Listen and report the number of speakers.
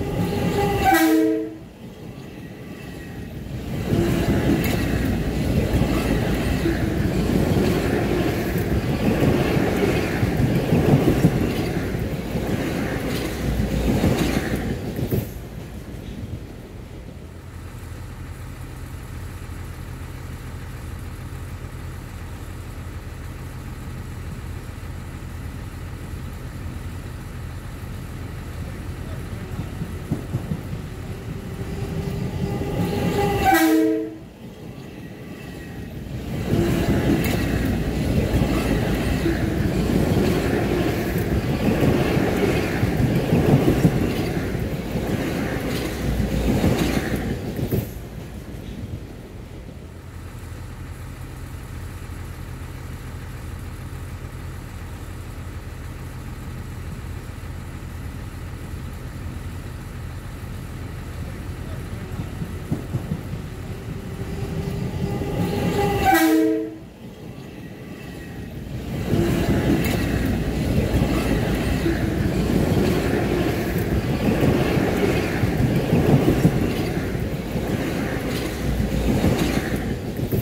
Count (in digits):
0